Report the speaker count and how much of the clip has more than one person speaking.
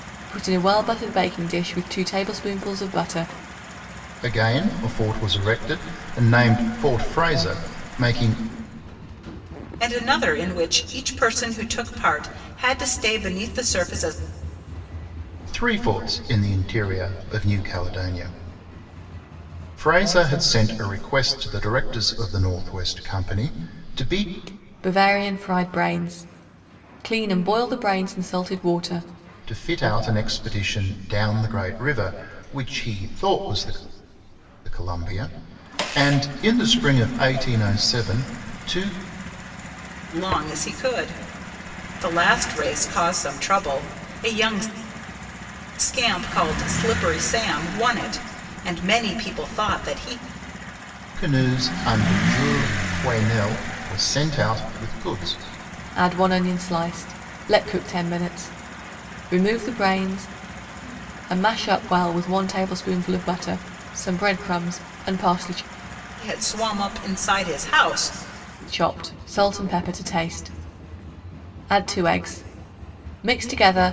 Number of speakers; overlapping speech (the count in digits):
3, no overlap